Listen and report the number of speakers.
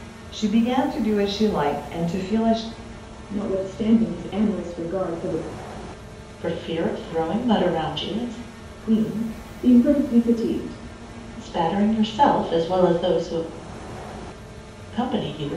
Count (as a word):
three